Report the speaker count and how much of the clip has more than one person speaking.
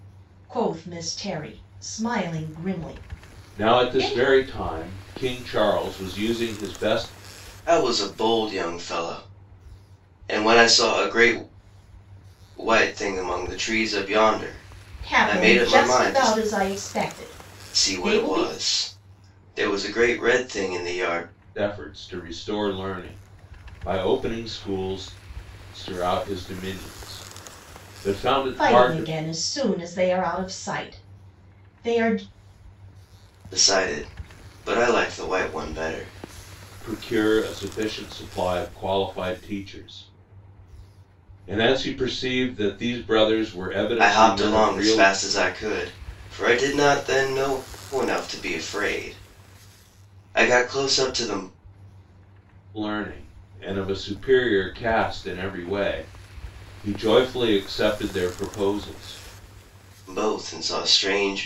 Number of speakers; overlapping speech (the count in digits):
3, about 7%